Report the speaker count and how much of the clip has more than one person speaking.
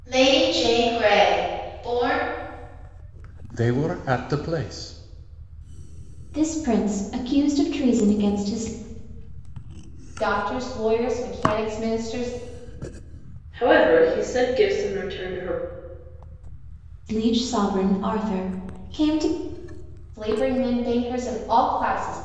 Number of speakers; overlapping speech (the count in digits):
5, no overlap